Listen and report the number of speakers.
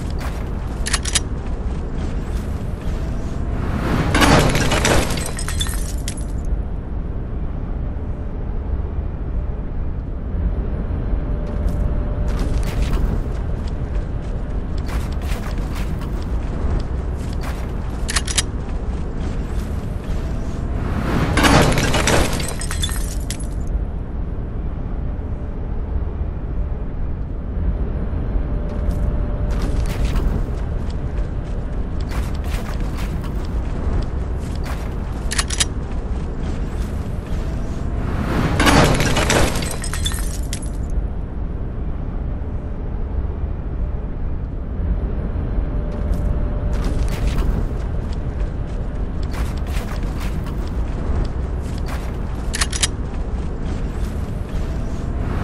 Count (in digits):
0